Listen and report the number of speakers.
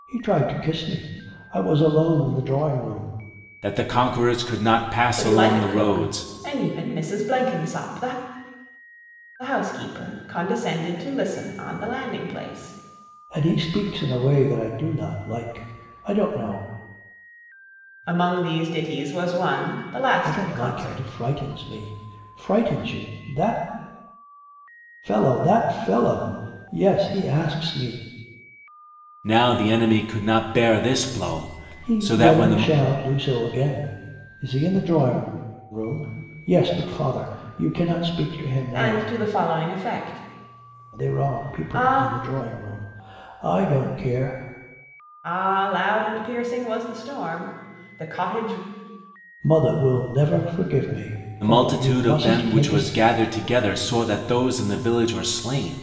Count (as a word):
three